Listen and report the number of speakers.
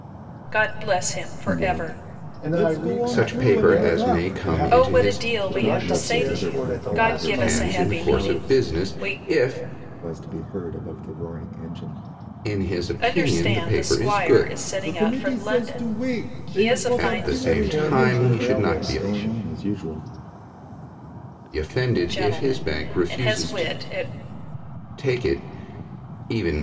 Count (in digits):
4